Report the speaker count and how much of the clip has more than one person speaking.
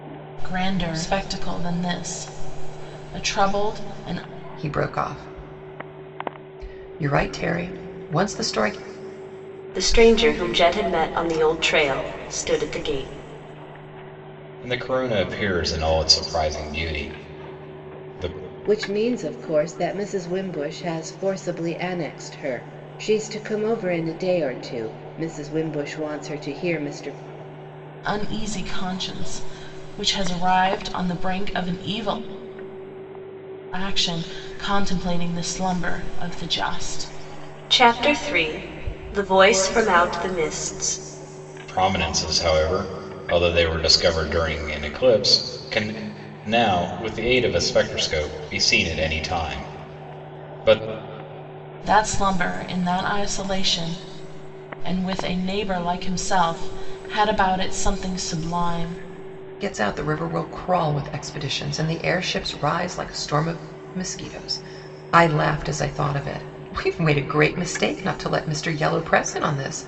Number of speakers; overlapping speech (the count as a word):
five, no overlap